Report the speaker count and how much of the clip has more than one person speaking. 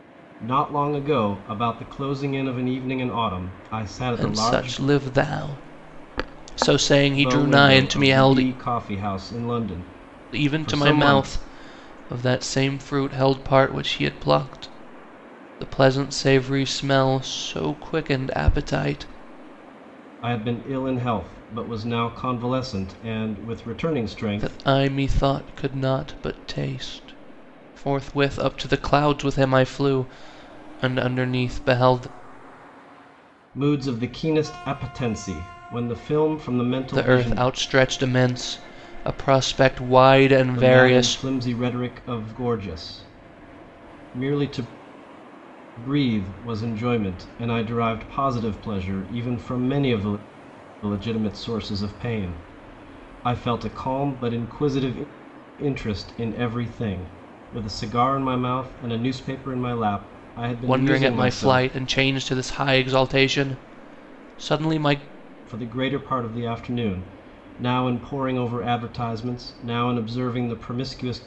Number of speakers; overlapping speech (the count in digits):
2, about 8%